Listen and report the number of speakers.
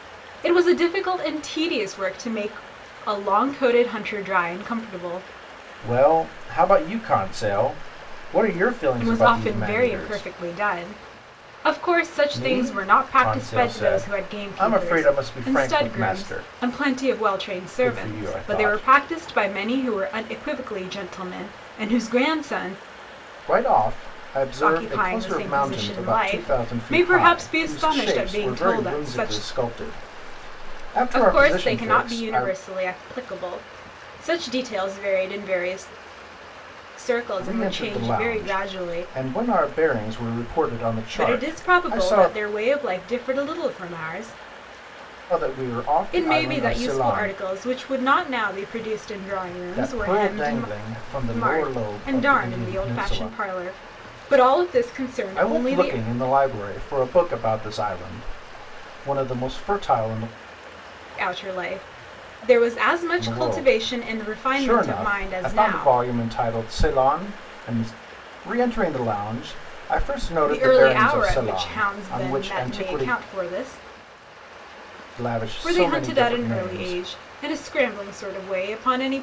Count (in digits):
2